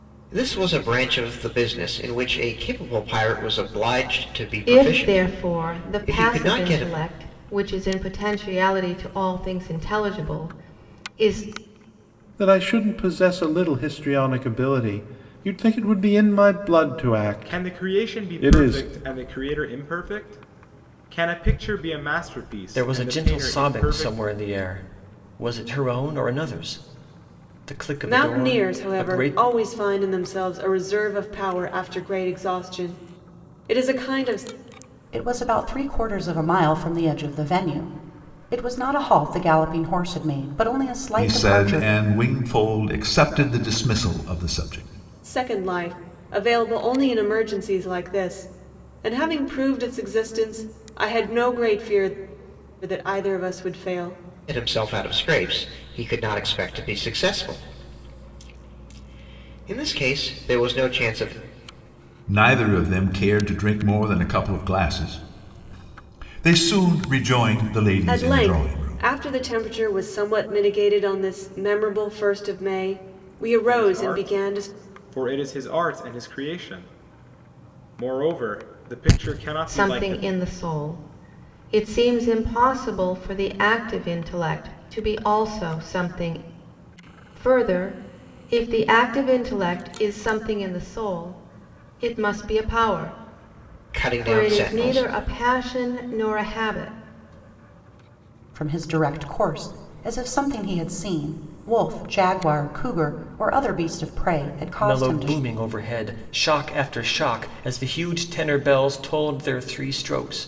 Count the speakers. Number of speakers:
8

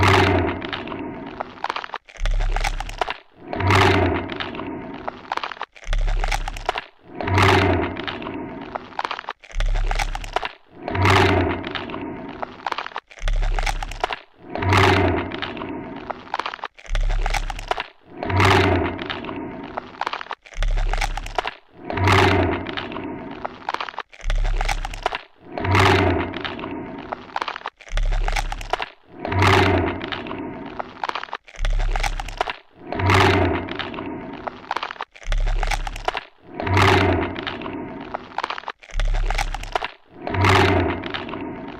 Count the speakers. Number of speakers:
0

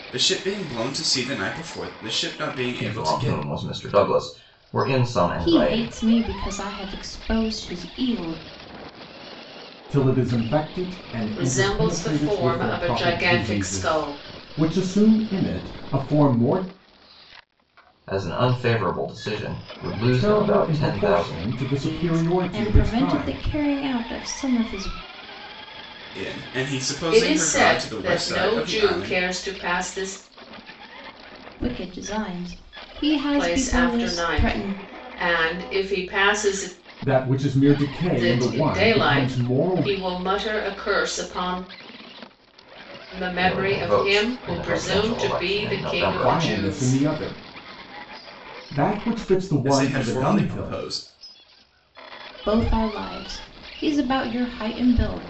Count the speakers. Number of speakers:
5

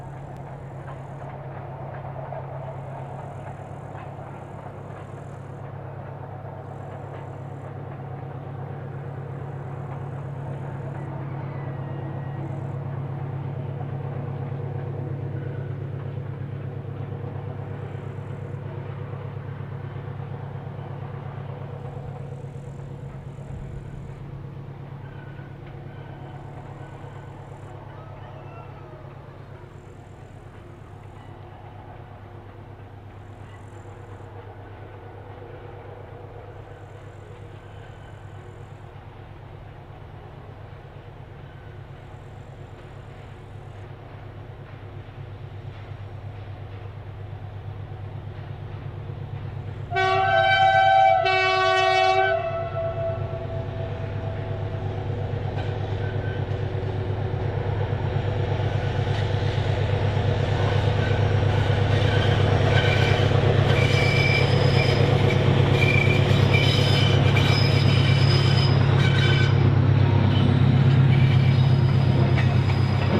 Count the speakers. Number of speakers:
0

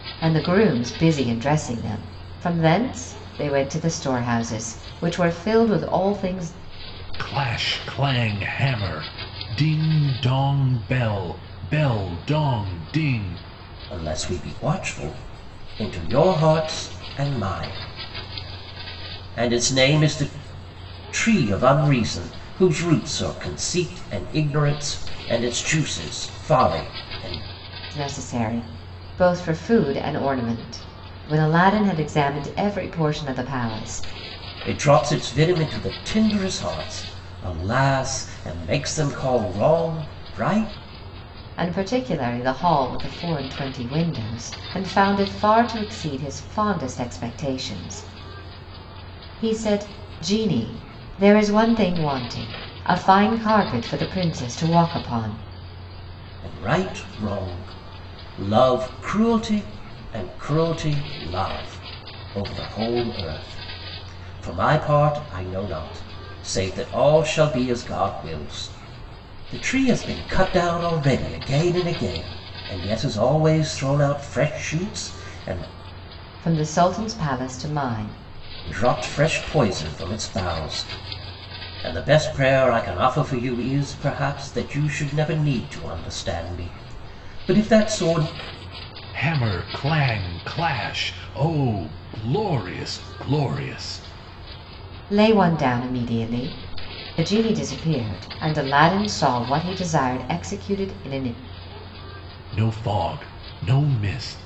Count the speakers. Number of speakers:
3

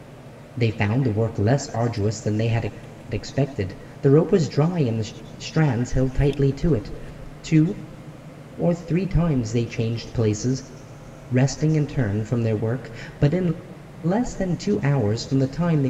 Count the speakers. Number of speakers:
1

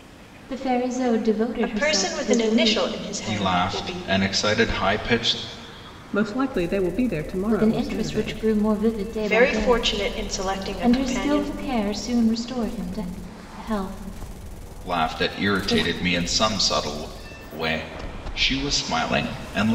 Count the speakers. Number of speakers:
4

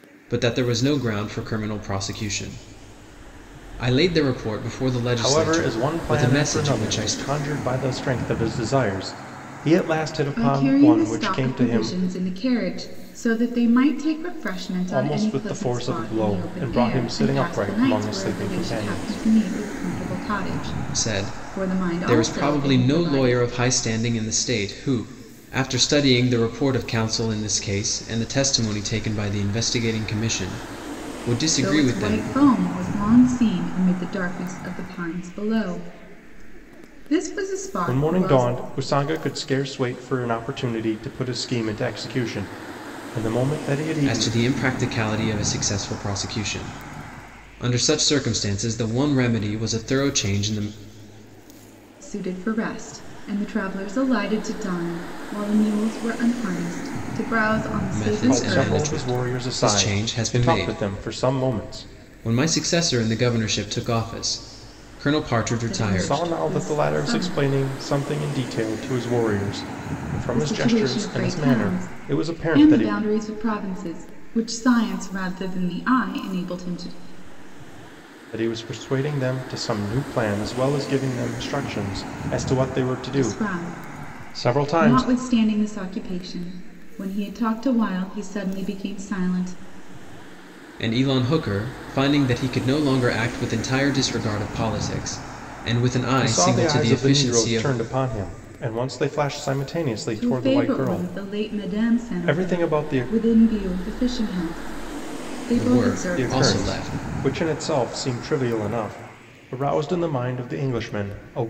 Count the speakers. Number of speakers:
3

